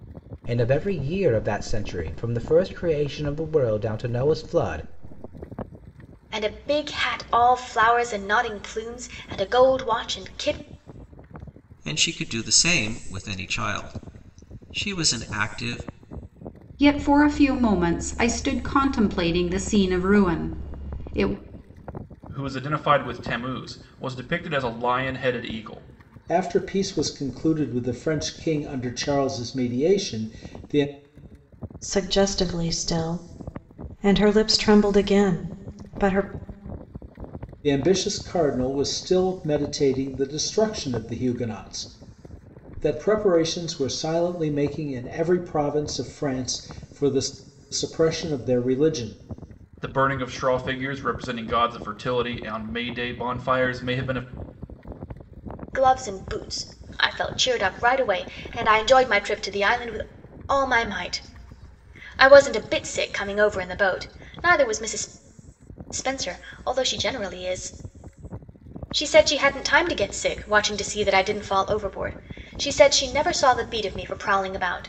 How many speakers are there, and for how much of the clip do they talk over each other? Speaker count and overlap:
7, no overlap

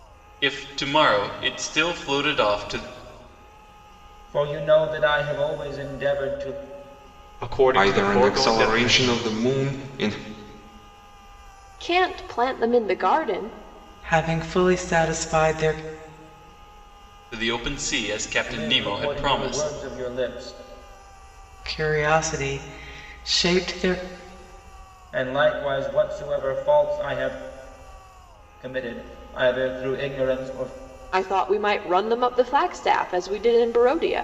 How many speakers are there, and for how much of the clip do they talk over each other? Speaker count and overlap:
6, about 8%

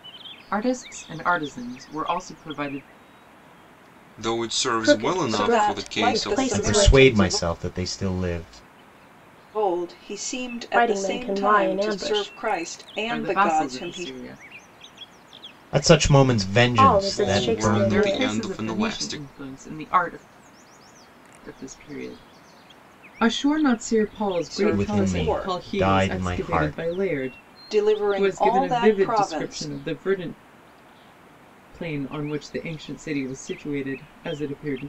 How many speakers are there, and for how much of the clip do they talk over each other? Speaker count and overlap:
5, about 34%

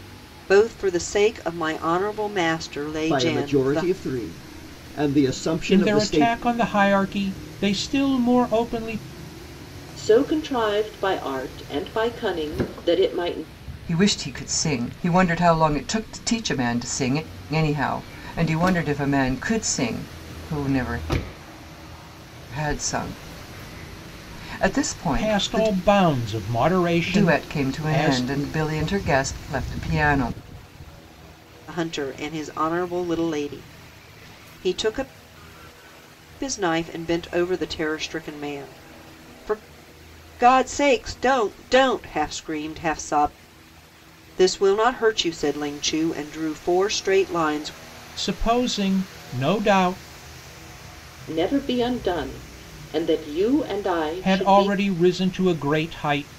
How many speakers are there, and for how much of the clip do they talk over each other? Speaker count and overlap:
5, about 7%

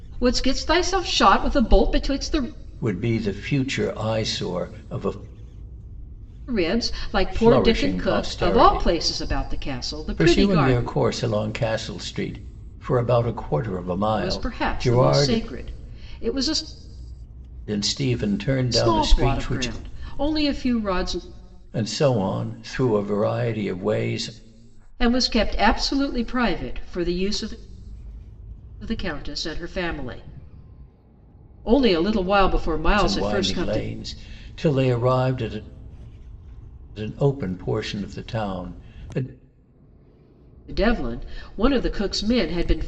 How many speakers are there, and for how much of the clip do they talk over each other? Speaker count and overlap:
2, about 13%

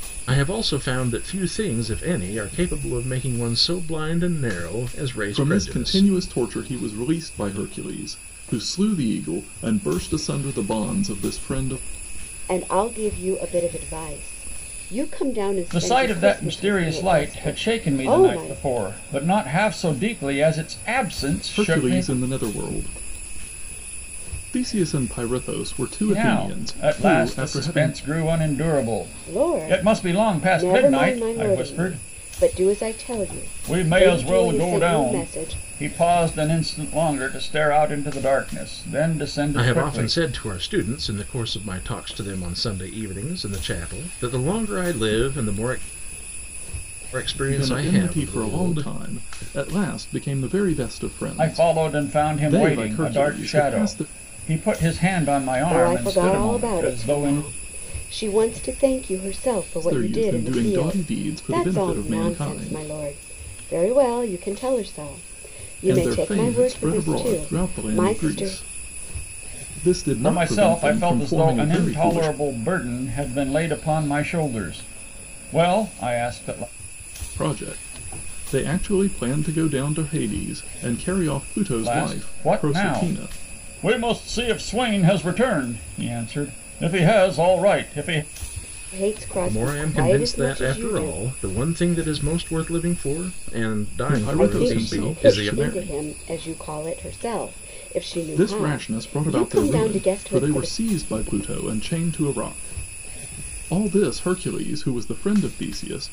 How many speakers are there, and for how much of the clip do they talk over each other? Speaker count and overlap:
4, about 31%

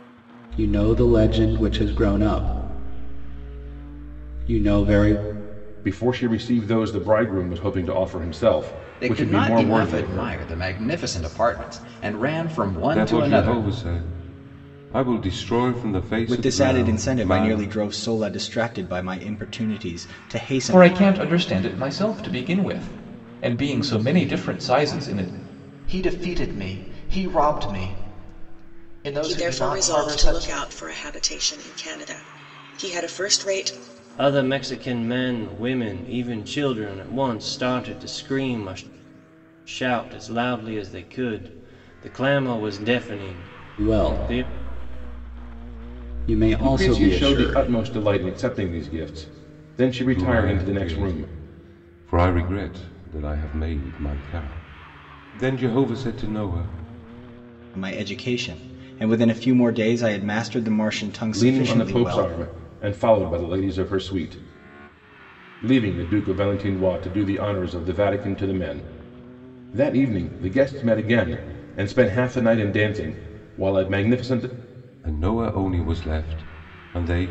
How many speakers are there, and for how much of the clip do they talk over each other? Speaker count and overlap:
9, about 12%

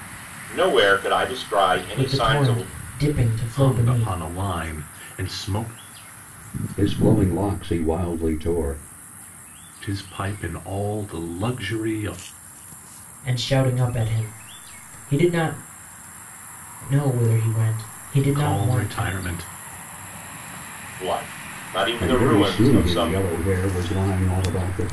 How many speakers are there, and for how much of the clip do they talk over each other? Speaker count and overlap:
4, about 14%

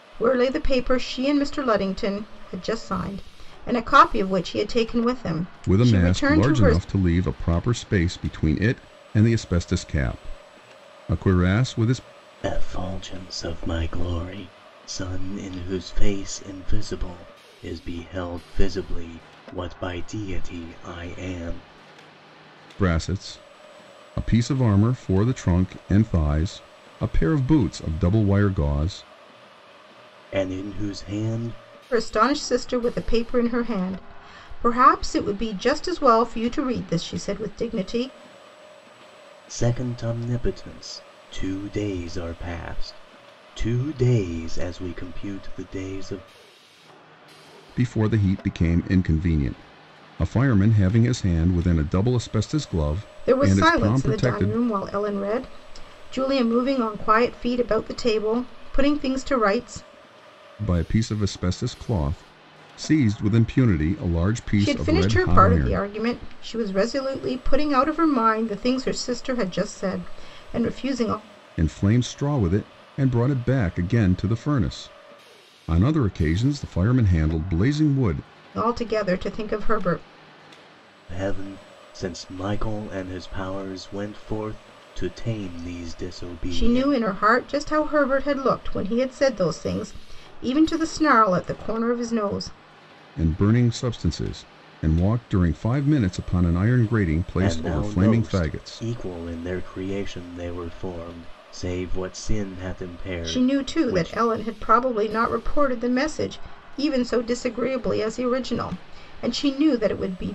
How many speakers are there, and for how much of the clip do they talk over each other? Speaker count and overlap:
3, about 6%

